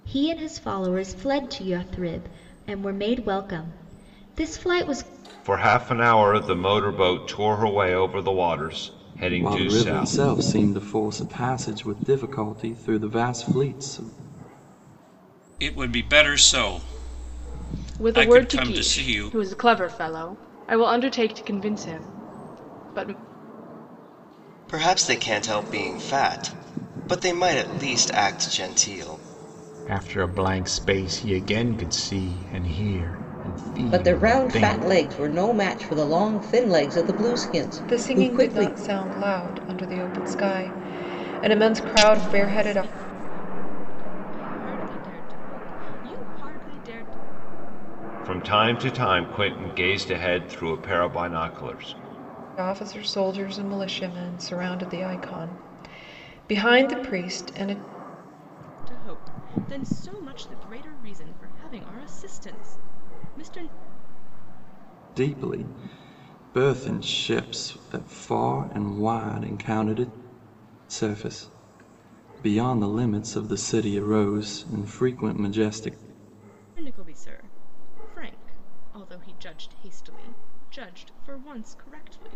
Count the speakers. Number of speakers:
10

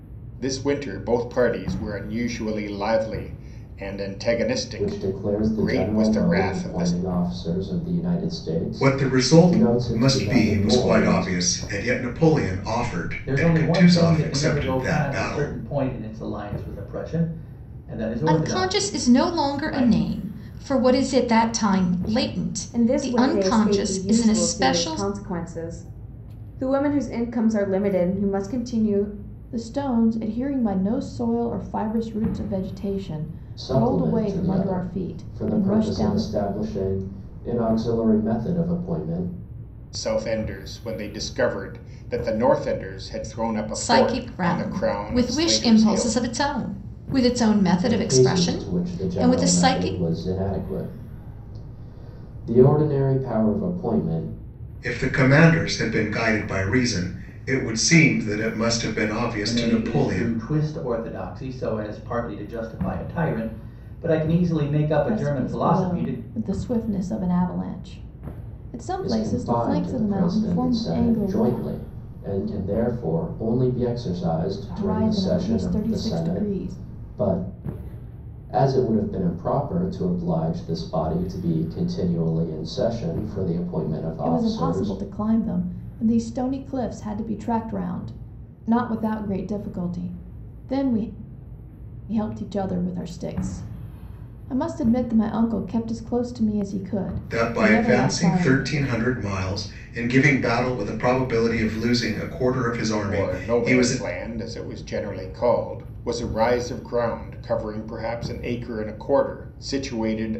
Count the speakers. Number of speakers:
7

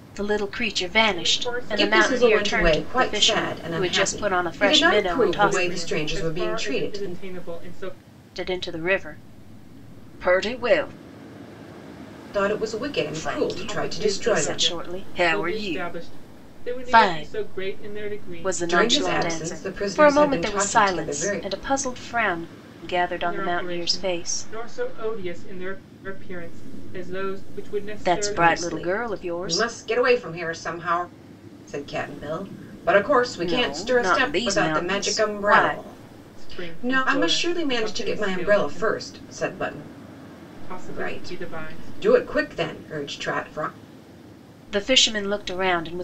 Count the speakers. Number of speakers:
3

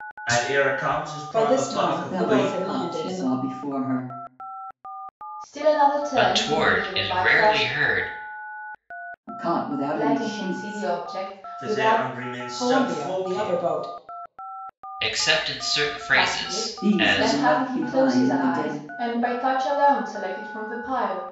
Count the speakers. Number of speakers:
5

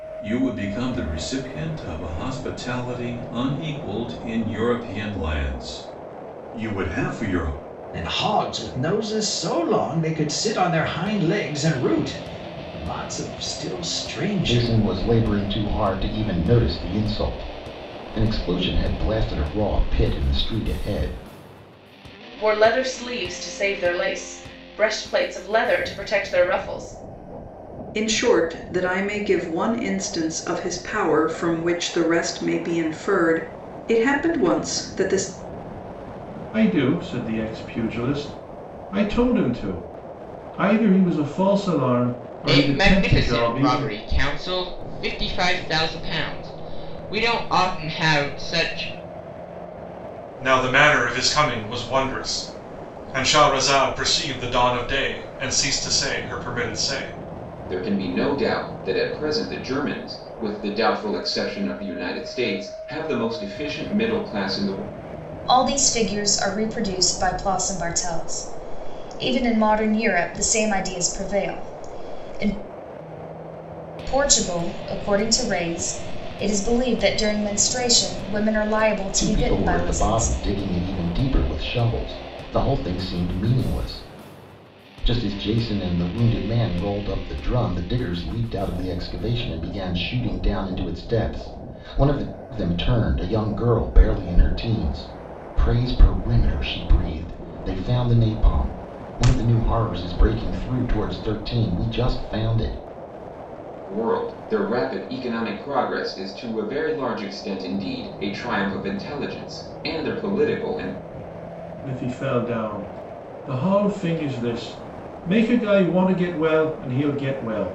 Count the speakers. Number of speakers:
10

